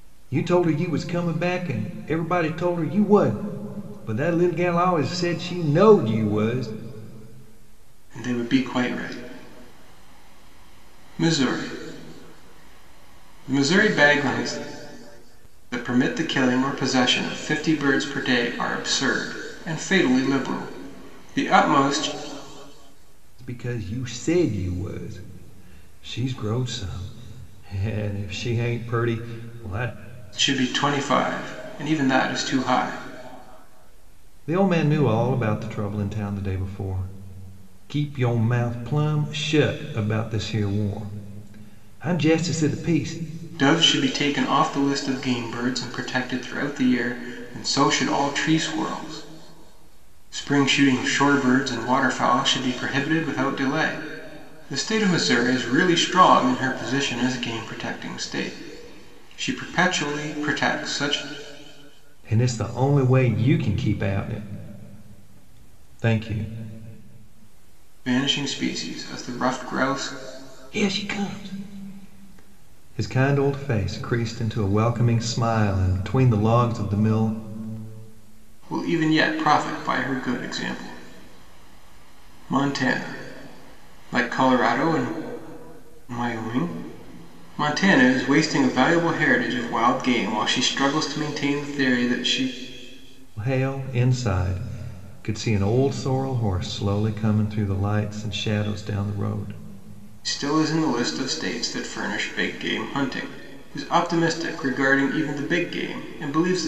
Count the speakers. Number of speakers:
two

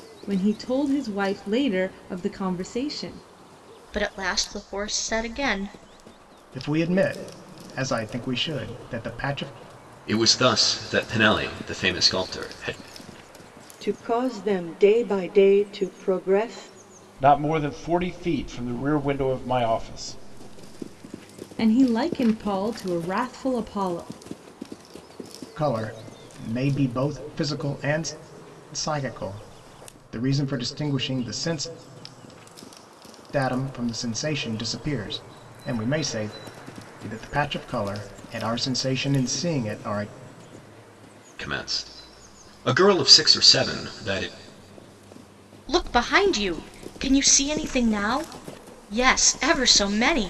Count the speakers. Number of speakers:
six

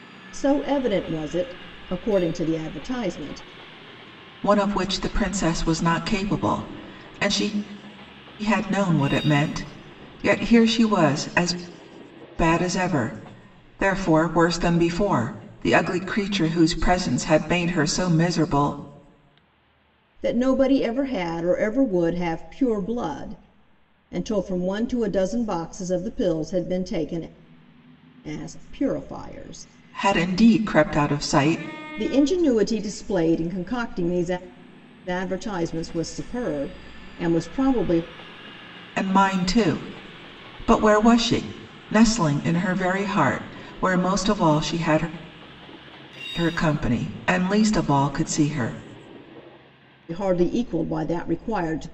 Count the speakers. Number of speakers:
two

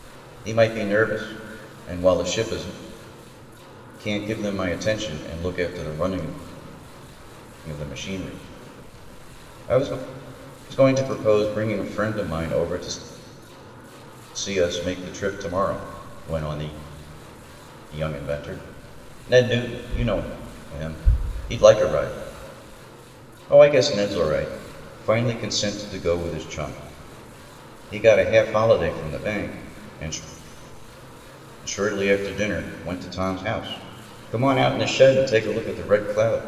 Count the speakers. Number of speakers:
one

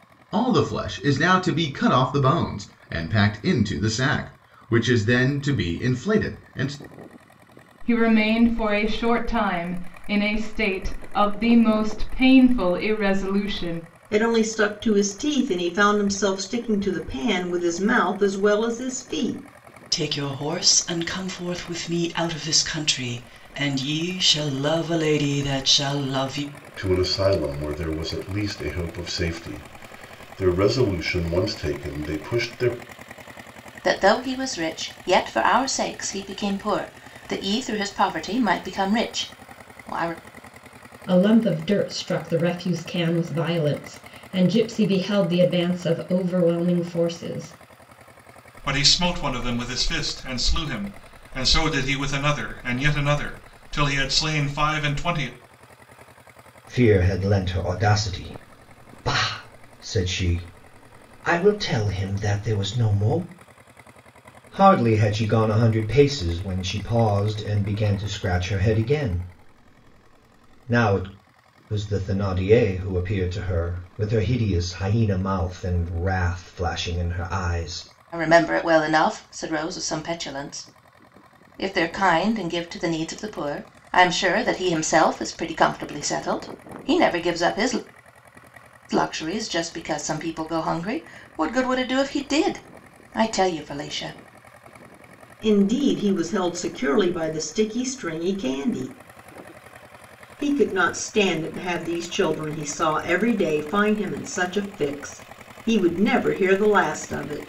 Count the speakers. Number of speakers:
nine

